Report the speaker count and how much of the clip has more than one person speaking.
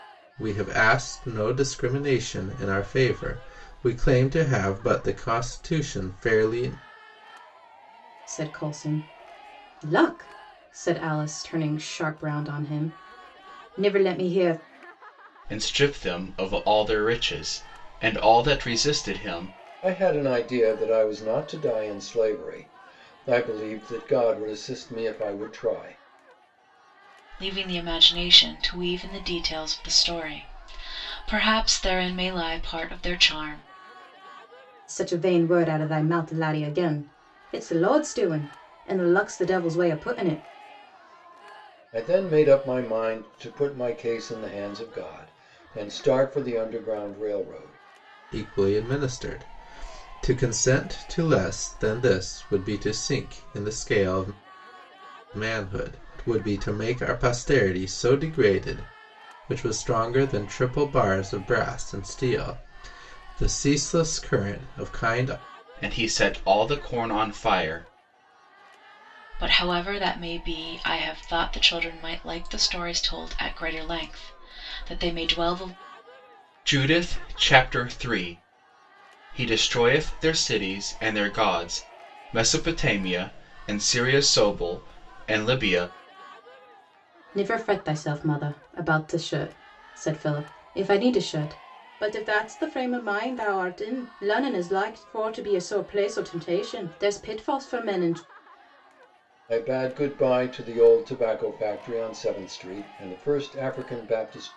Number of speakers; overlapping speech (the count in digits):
5, no overlap